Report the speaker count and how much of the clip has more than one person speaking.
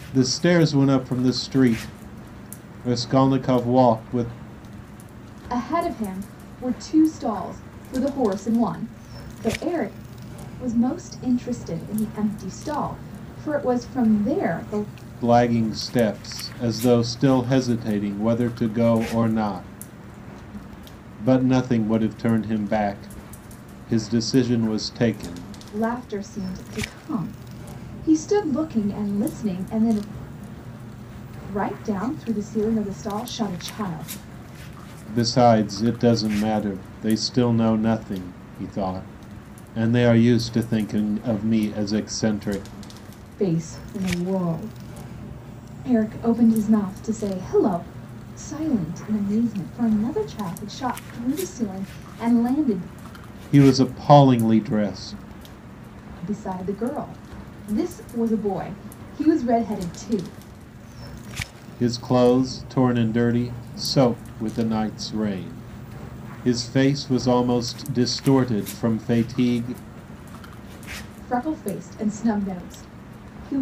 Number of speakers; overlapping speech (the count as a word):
two, no overlap